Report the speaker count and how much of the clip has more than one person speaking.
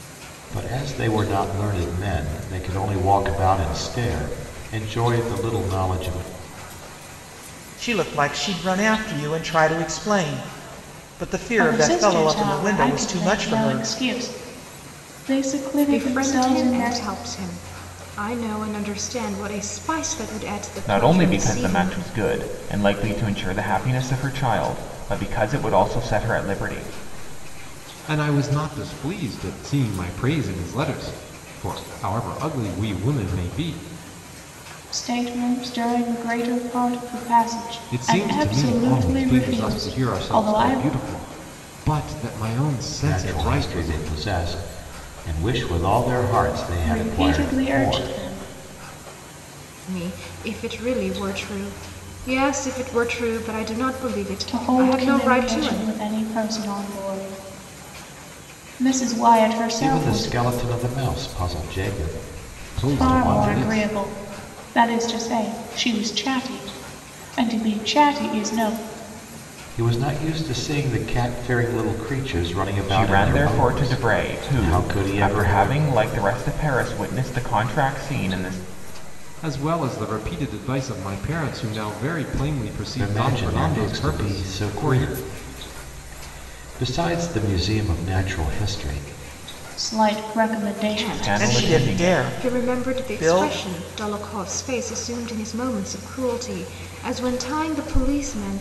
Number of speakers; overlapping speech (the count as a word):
six, about 21%